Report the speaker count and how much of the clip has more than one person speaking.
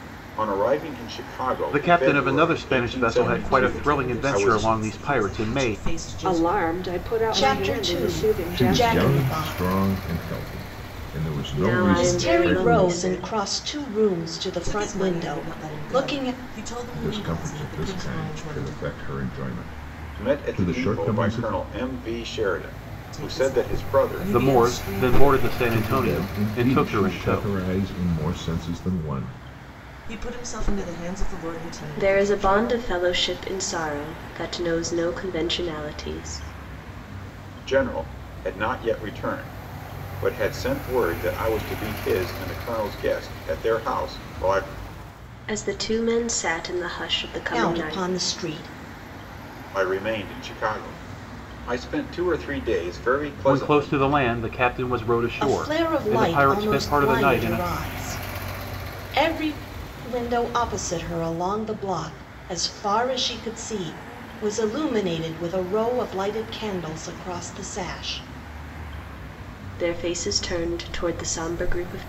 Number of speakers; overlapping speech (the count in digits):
7, about 32%